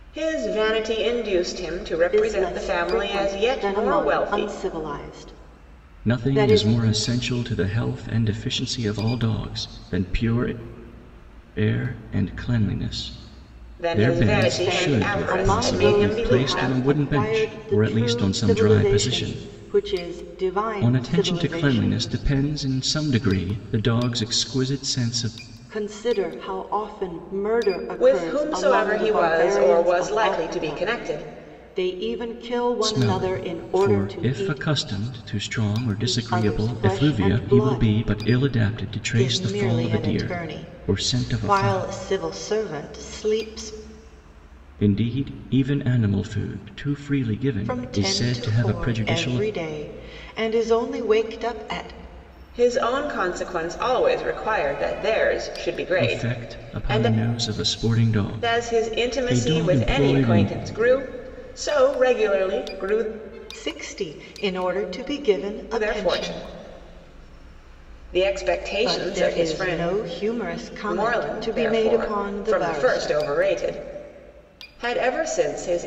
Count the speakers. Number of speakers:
3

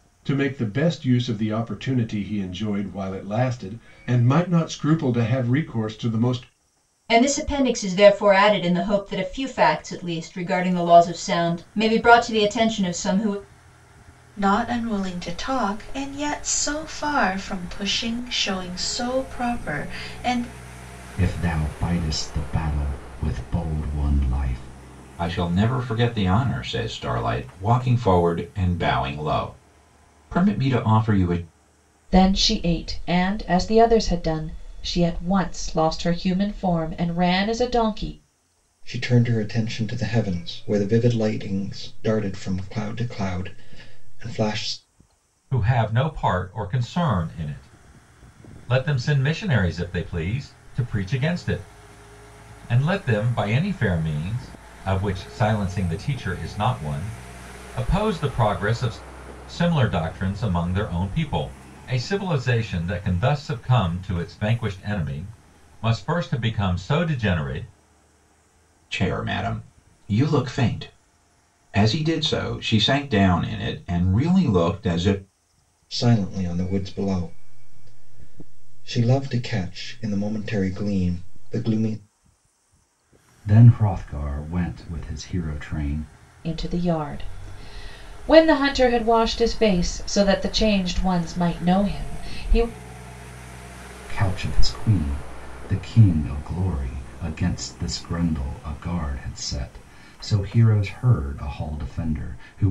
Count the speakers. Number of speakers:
8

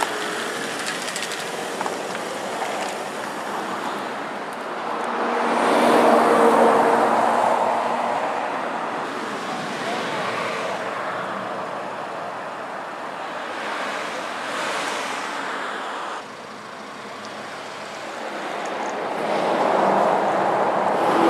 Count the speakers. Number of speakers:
0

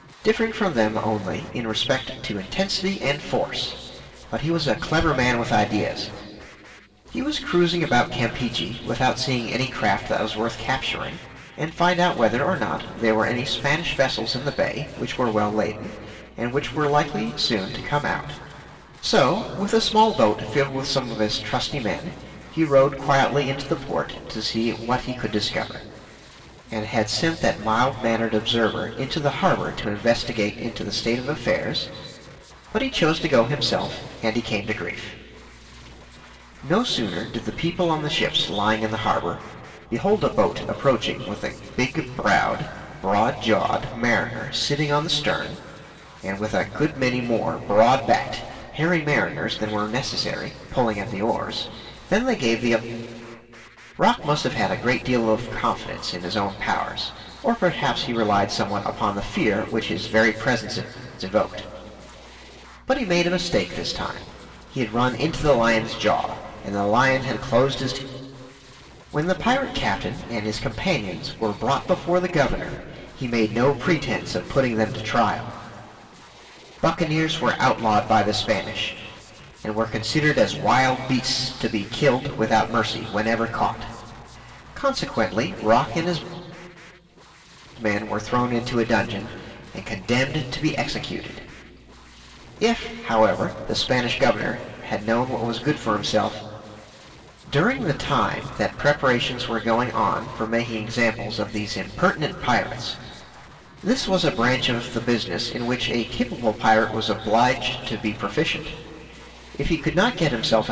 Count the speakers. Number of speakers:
1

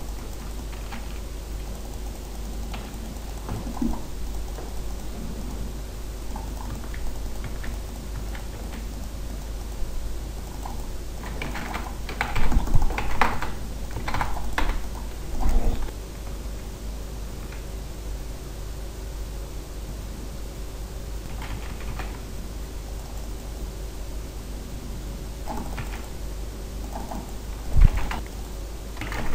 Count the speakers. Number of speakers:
0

